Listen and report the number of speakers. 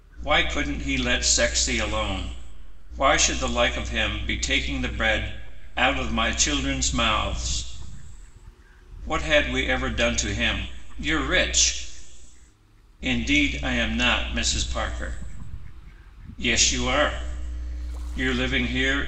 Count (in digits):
1